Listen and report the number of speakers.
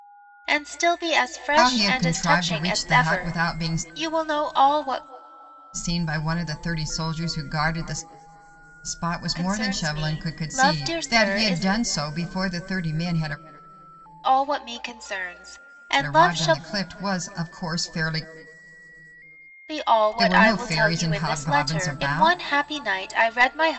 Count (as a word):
two